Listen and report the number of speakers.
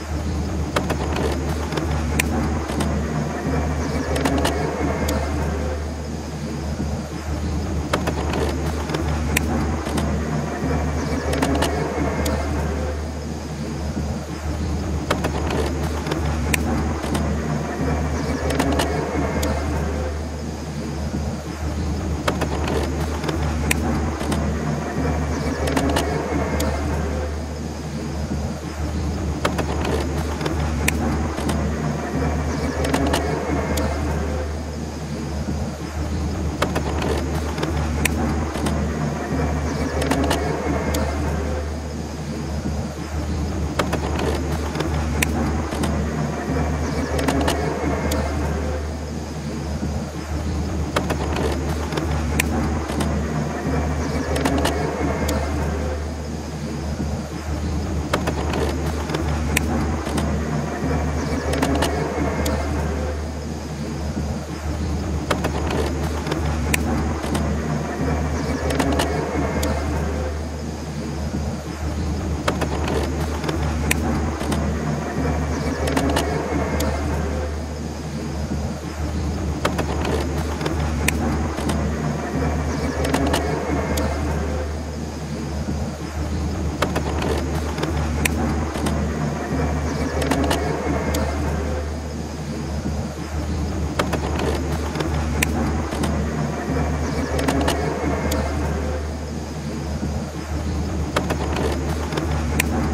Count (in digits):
0